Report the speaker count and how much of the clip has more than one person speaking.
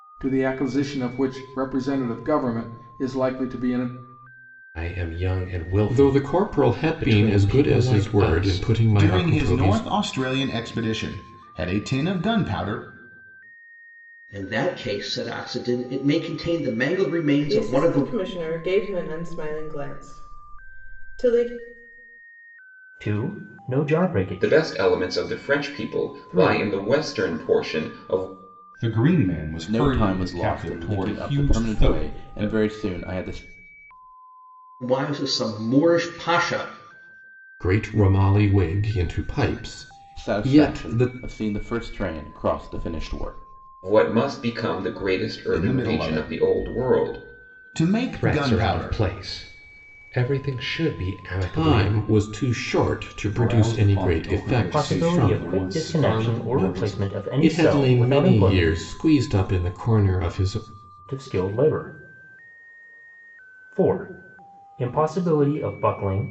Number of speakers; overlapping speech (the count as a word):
ten, about 29%